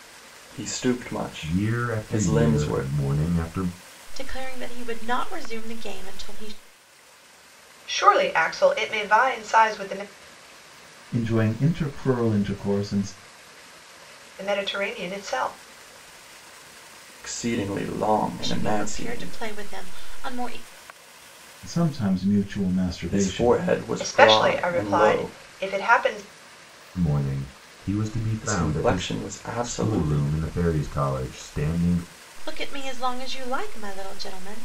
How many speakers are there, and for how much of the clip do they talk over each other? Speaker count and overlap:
5, about 17%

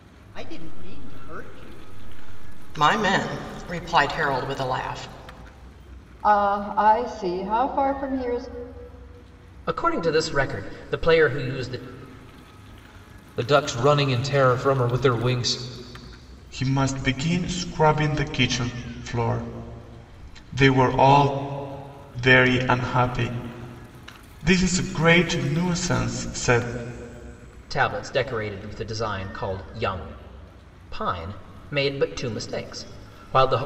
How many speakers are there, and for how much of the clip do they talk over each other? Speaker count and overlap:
6, no overlap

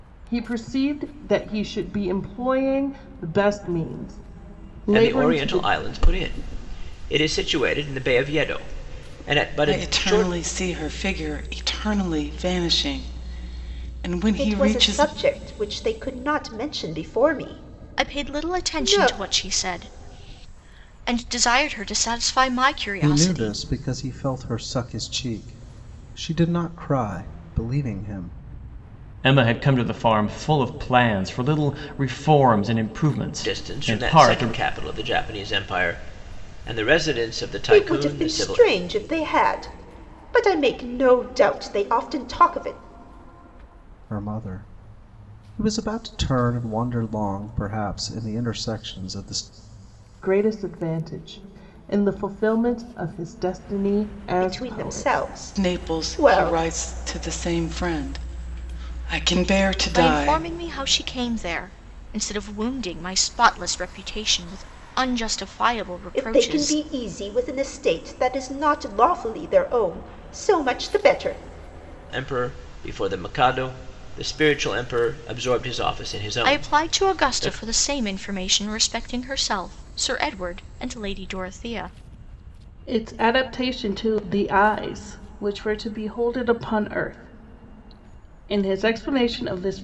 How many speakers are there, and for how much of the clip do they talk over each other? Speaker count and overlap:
7, about 12%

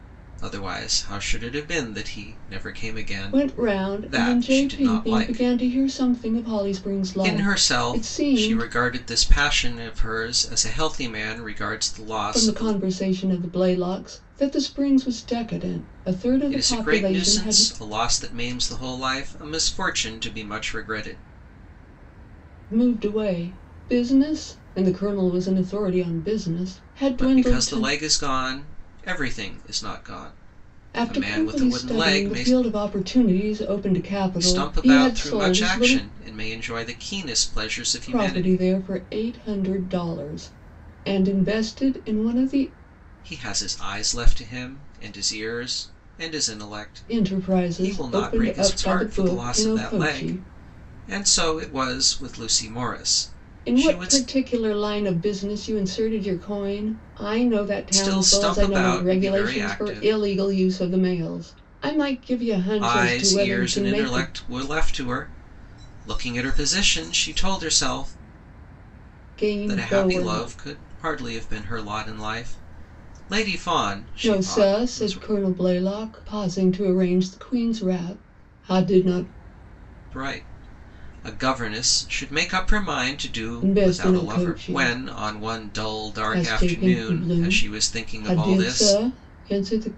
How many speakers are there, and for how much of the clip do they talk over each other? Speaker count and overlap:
2, about 27%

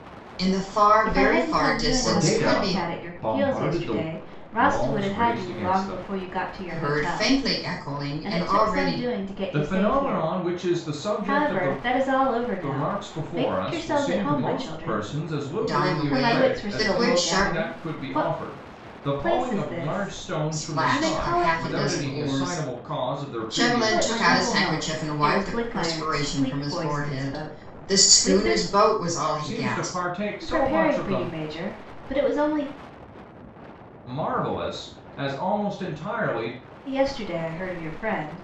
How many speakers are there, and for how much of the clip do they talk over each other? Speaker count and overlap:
3, about 60%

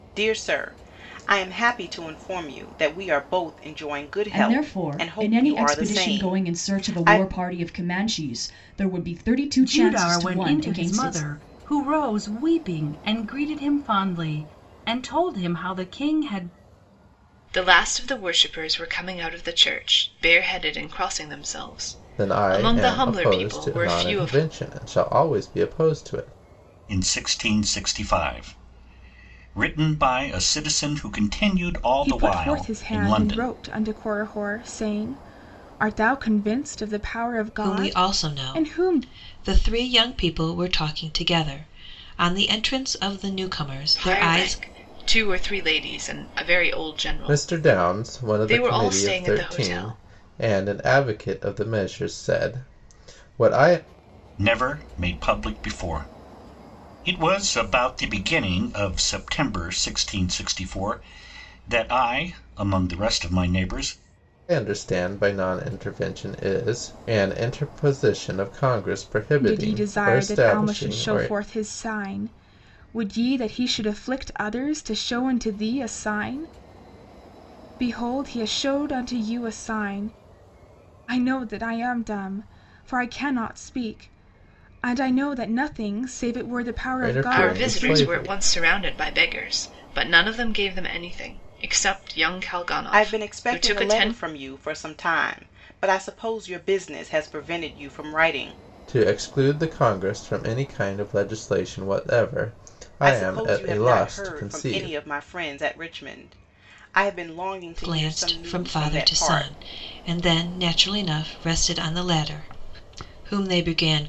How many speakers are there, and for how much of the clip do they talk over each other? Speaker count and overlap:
8, about 19%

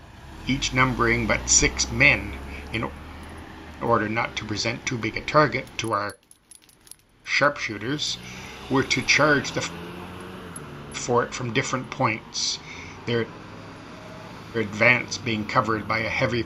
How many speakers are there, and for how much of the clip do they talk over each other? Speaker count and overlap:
1, no overlap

